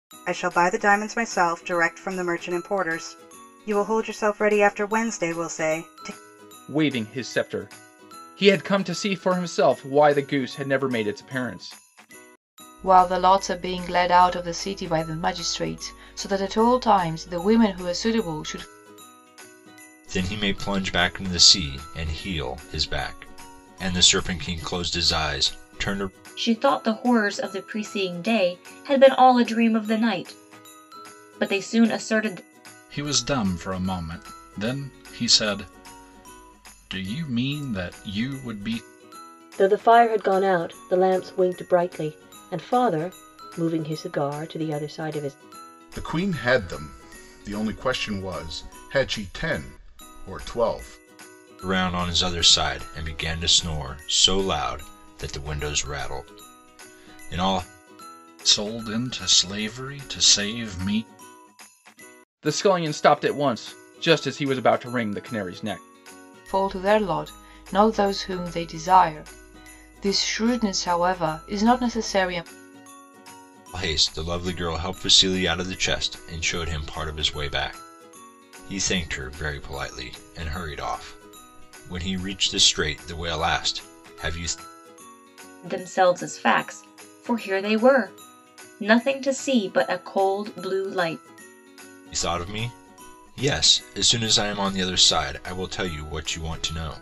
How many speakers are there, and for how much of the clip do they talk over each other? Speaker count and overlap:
8, no overlap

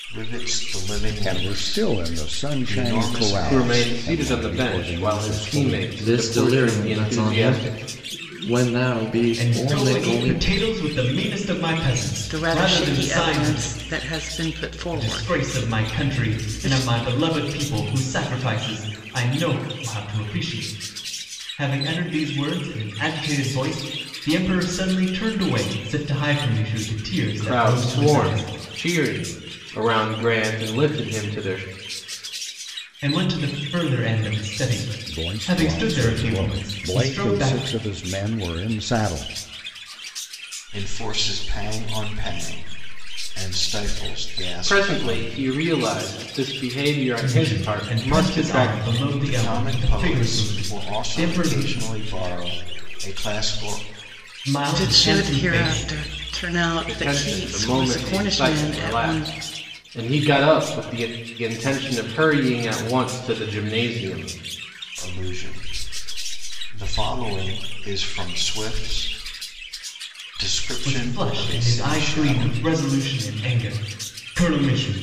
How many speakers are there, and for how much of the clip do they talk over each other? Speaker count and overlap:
6, about 33%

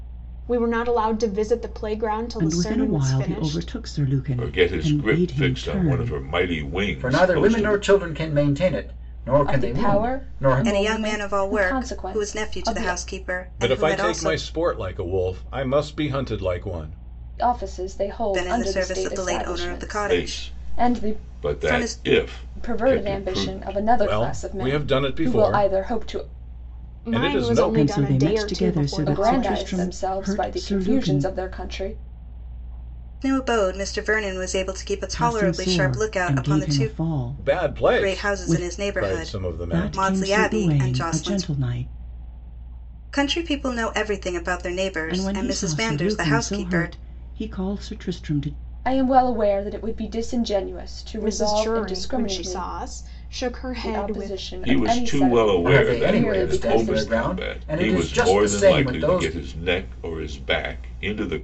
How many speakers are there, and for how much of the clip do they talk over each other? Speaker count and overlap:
7, about 57%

